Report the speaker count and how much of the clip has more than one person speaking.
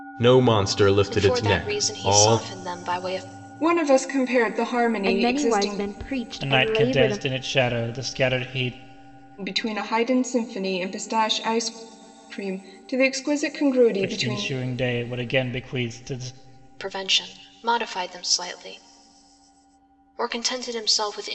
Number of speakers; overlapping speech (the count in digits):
5, about 17%